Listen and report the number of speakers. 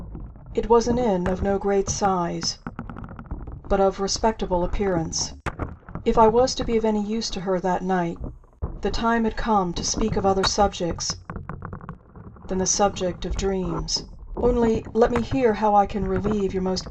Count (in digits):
1